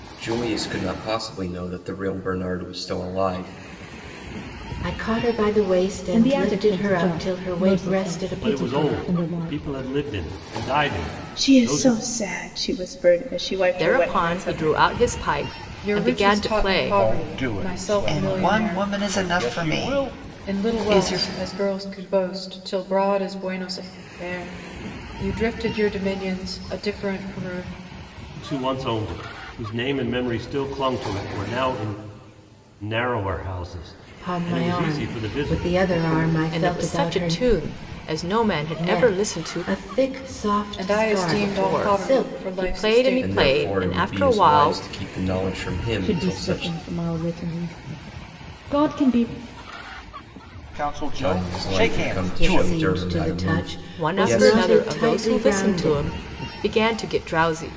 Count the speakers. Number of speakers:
9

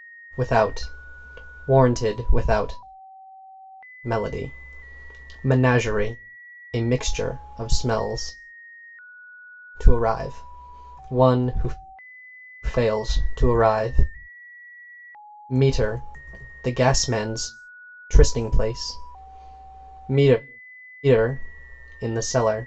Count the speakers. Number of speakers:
1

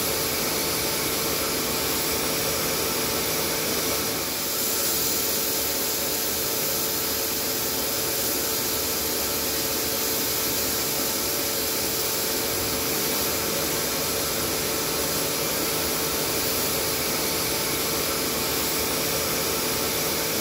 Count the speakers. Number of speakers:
0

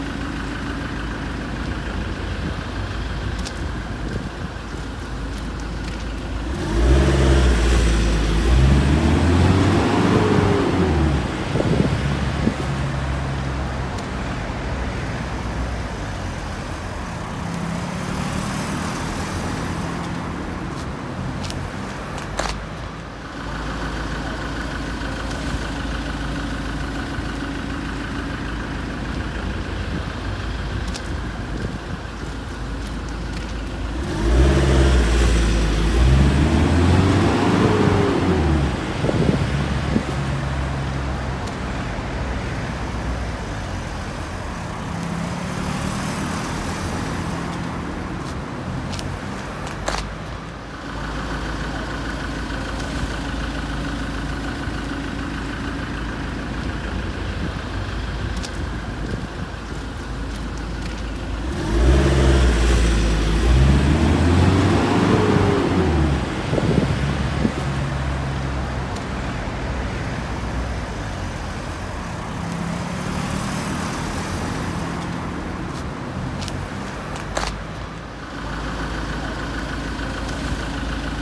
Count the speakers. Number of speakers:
0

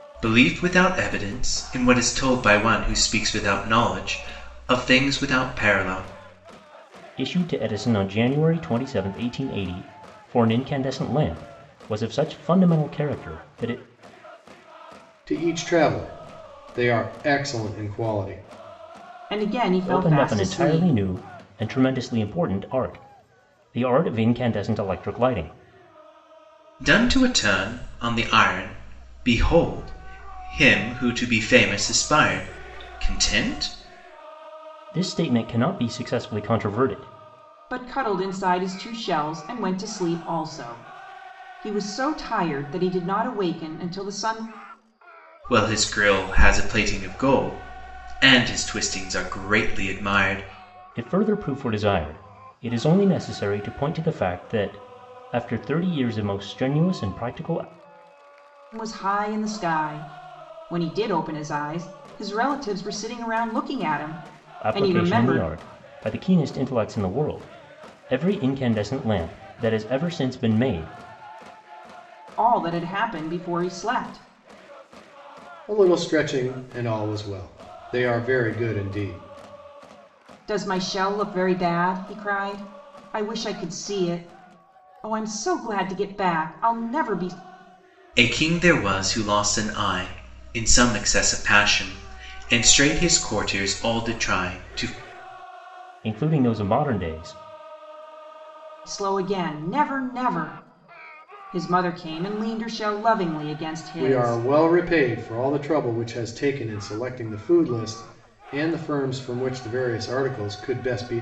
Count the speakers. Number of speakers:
4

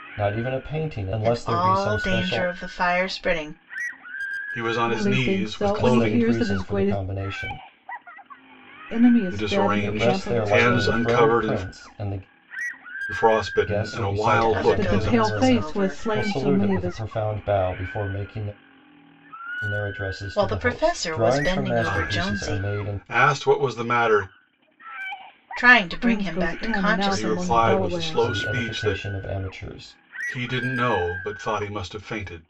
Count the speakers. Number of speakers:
4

